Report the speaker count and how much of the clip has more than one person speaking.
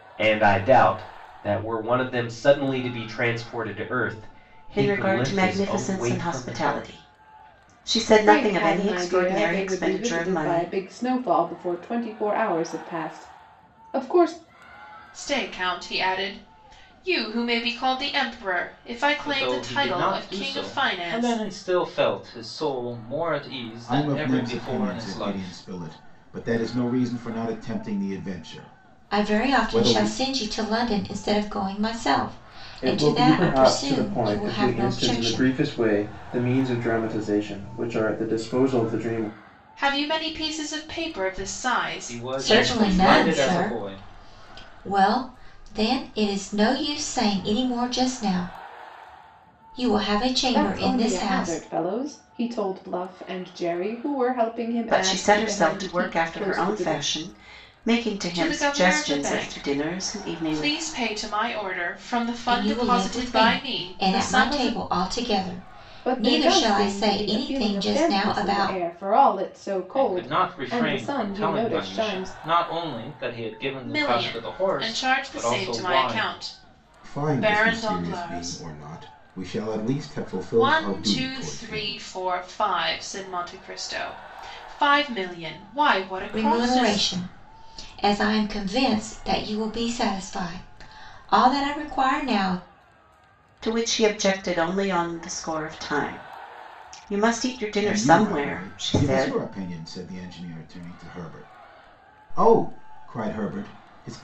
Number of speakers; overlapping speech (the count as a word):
eight, about 34%